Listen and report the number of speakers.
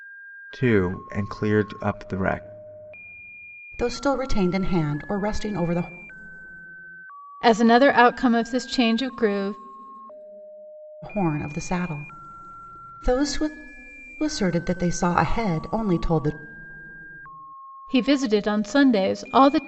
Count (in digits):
3